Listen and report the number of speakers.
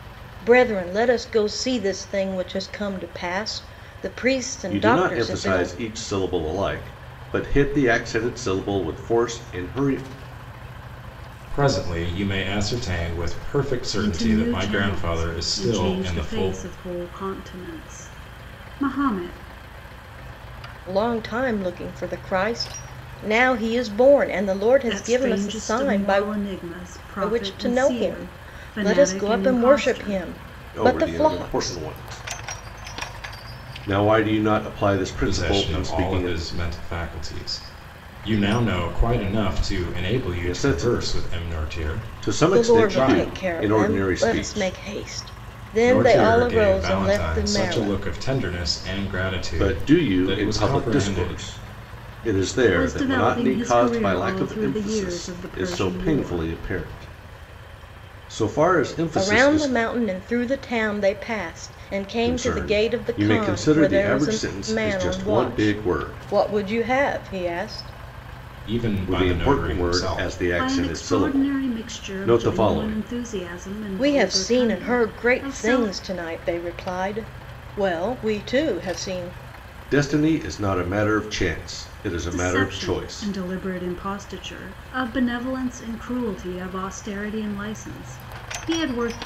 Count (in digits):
4